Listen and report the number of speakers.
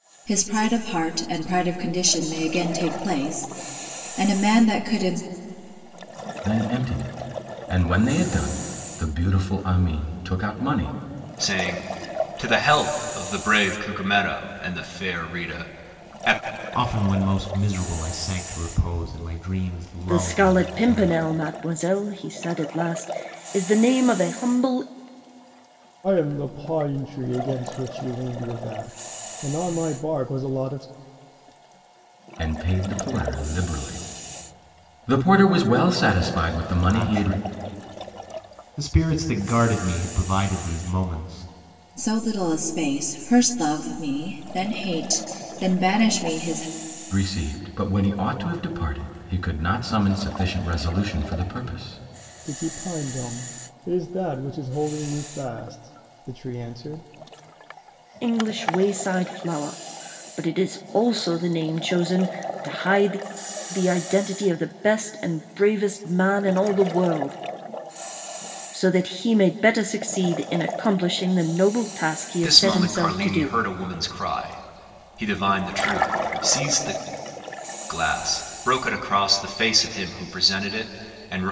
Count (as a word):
six